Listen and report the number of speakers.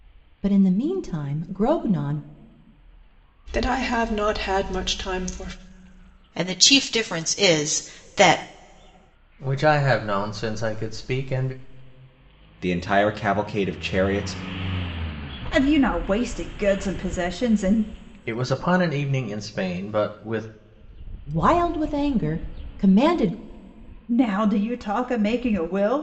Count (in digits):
6